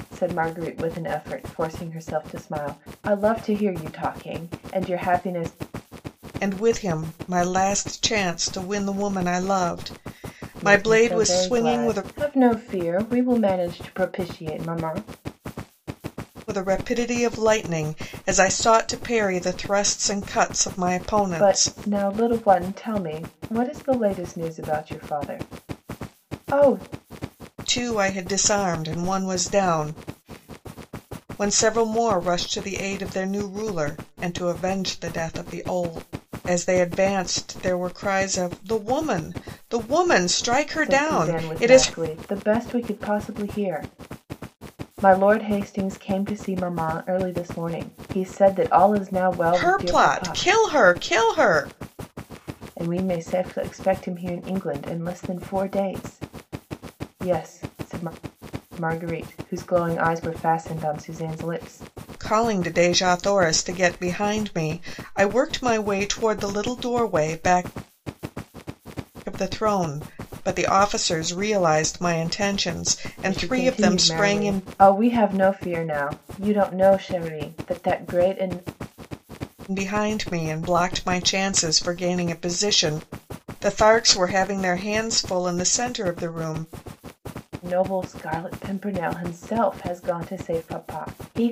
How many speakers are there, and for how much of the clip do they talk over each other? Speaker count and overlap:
two, about 6%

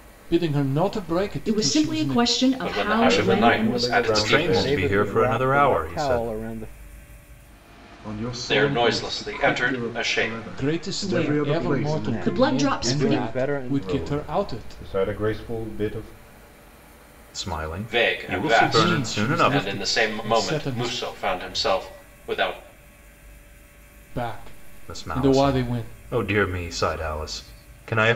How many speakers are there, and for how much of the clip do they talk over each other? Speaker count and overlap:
seven, about 55%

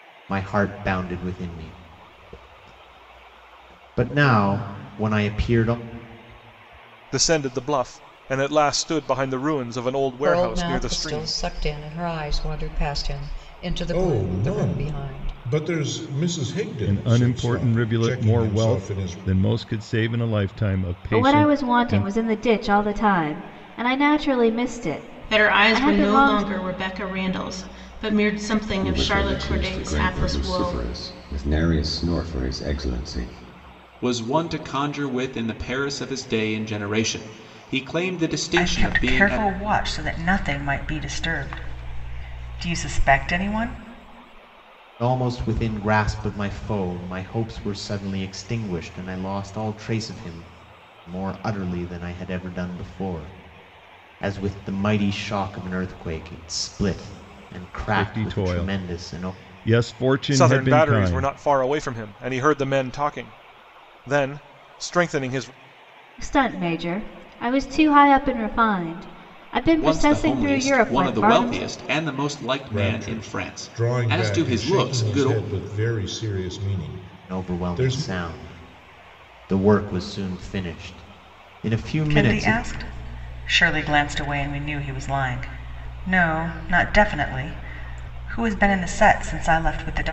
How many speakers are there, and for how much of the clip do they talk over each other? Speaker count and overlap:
ten, about 21%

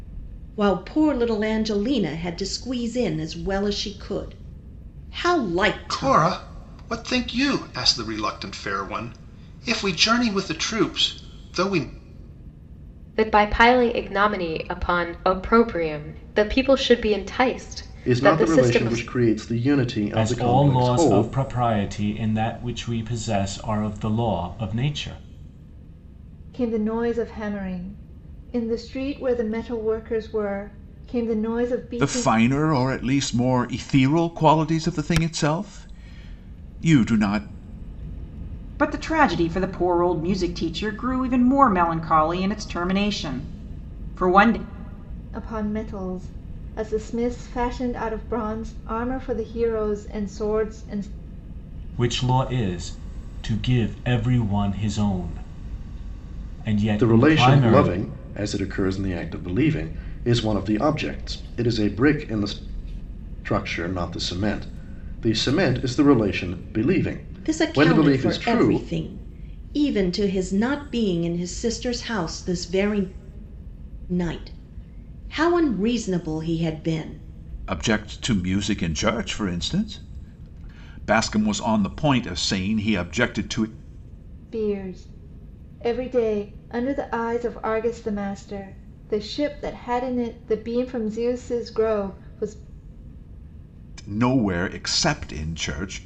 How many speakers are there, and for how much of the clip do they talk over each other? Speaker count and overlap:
eight, about 6%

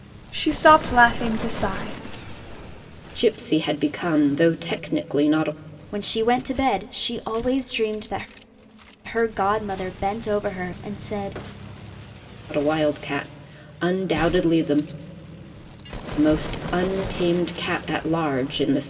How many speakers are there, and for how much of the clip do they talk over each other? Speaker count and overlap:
three, no overlap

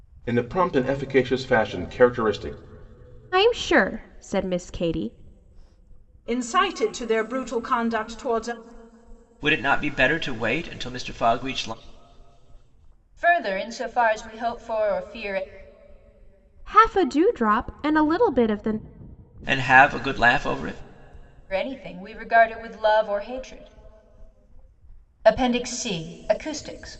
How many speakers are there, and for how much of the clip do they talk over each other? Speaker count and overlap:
five, no overlap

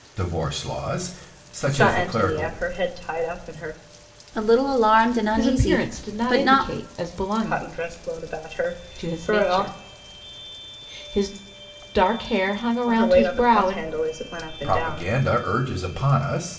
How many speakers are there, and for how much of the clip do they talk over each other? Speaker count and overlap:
four, about 31%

